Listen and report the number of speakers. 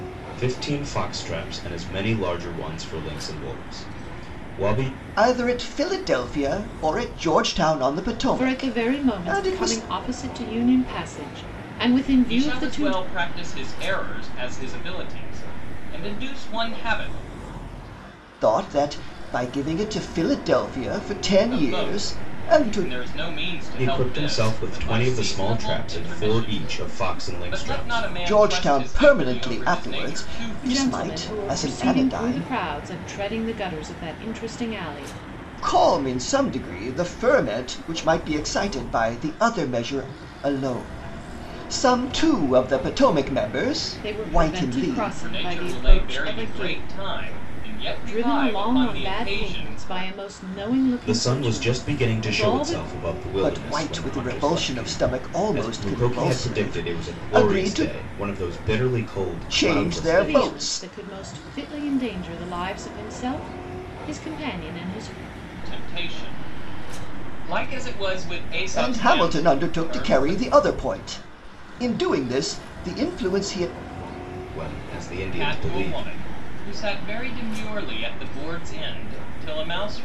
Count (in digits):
4